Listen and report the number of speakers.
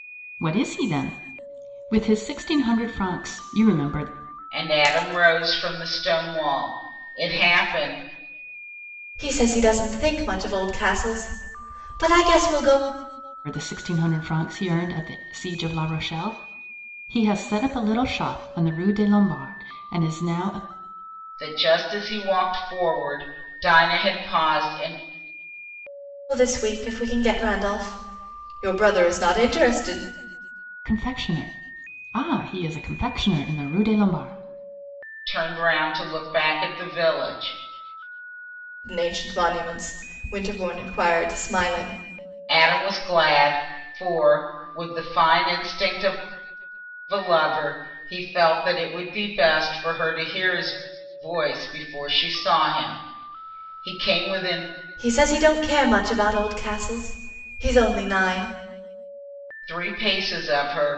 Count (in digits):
3